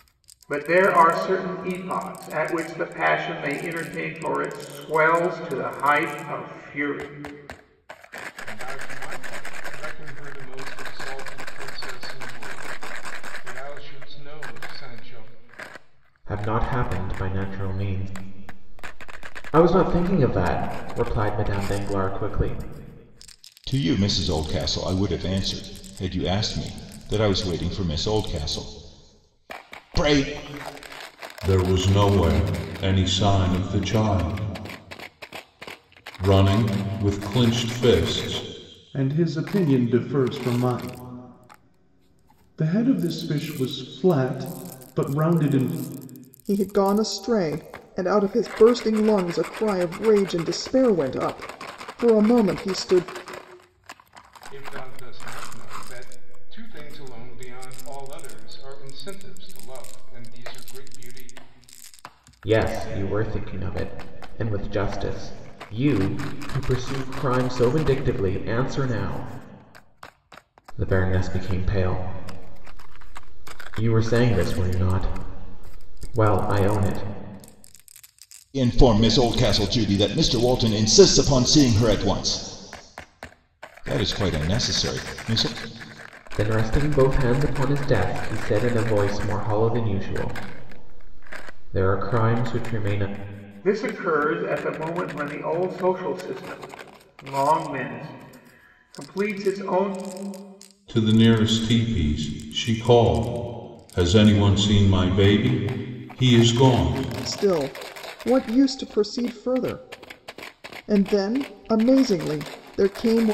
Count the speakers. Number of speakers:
7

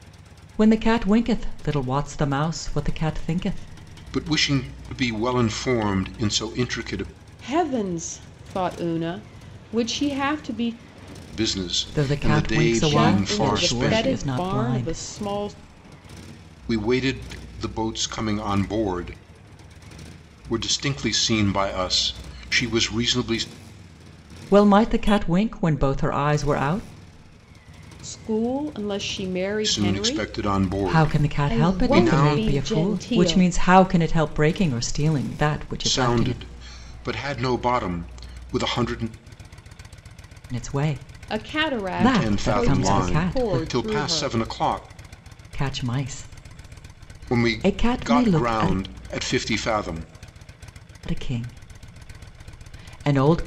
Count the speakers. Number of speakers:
3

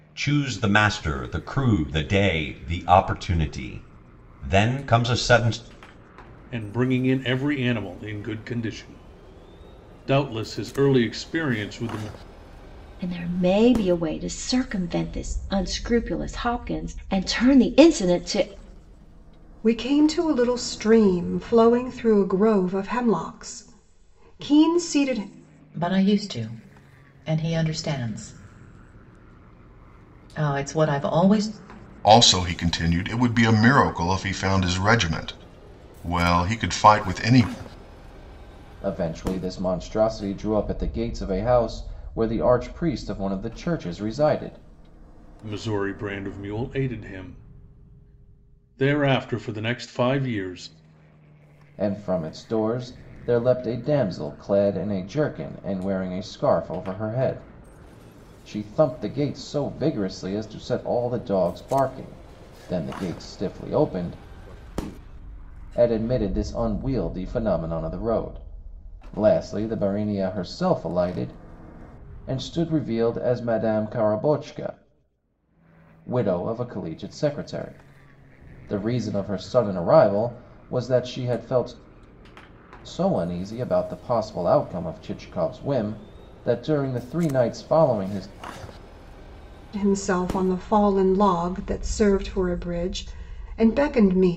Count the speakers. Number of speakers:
7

